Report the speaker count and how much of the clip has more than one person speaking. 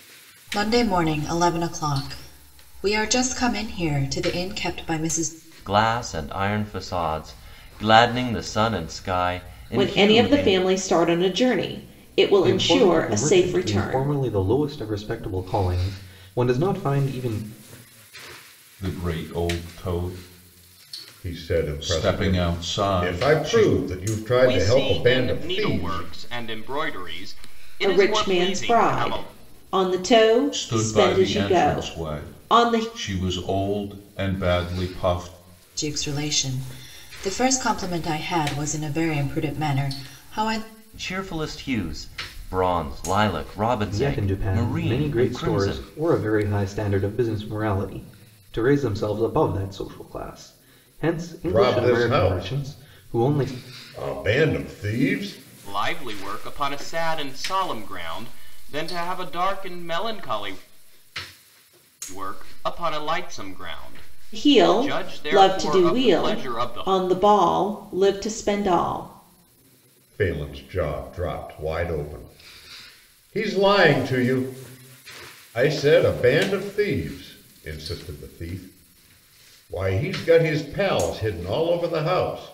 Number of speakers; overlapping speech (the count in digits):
7, about 21%